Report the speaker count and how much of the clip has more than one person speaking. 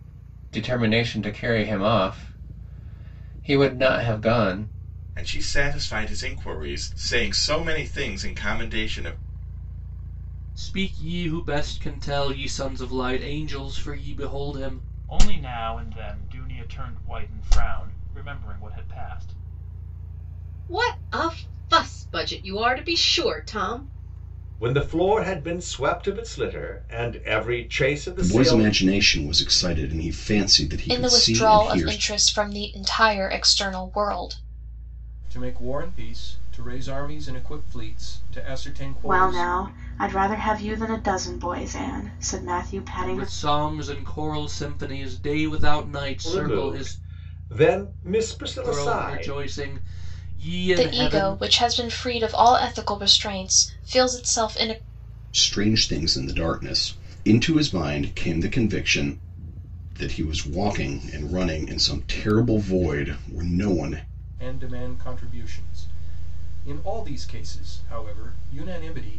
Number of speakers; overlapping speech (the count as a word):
ten, about 7%